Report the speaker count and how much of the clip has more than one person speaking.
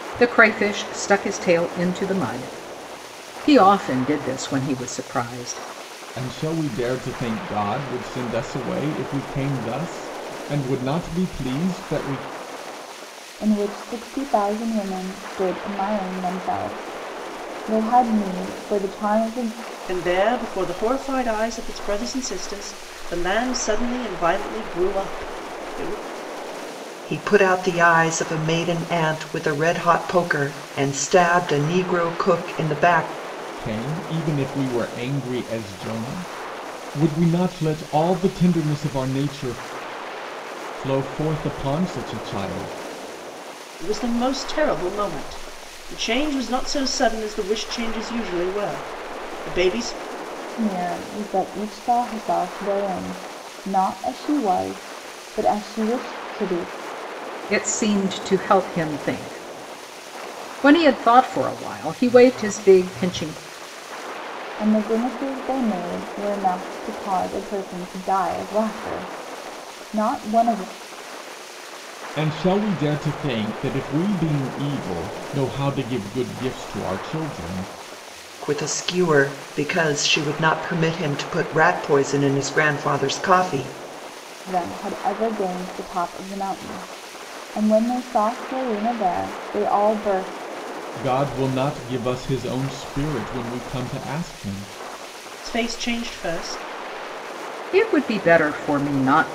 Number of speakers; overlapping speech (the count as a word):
five, no overlap